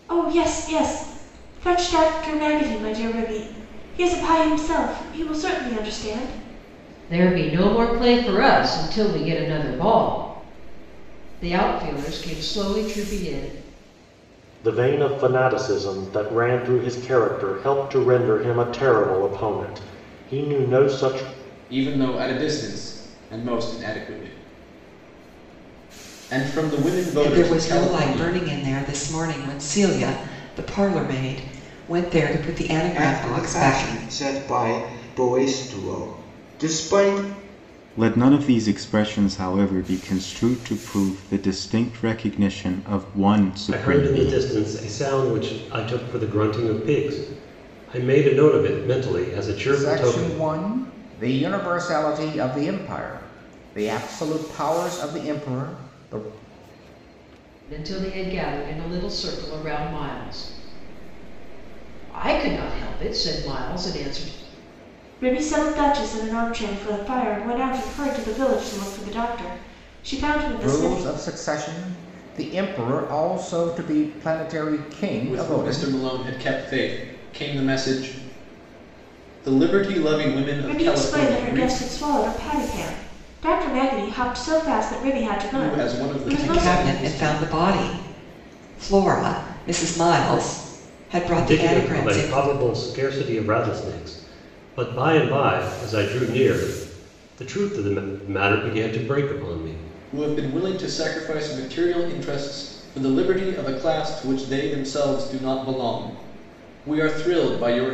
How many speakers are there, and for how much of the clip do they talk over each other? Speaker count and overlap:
nine, about 9%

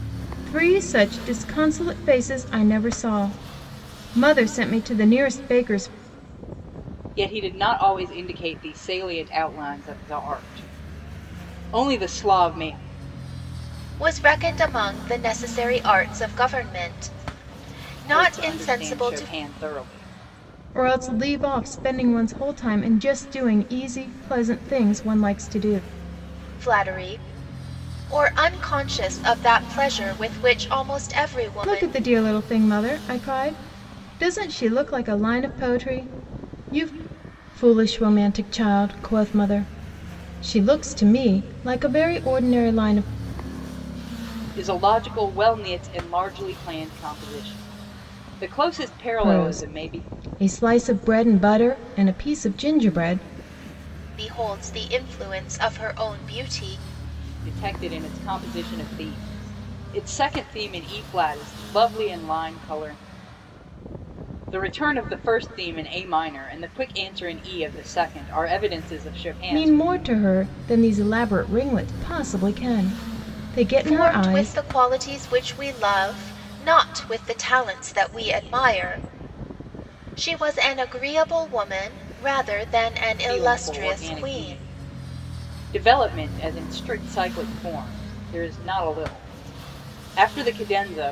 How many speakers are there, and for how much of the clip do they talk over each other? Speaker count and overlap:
three, about 6%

